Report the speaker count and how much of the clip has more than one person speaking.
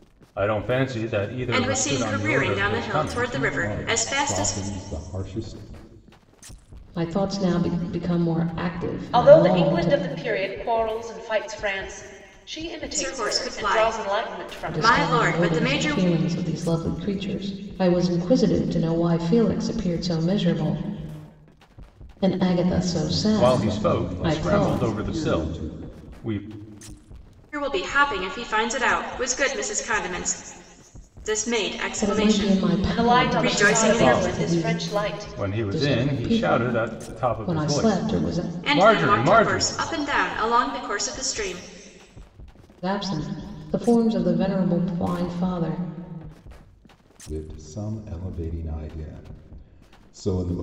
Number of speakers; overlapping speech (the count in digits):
5, about 34%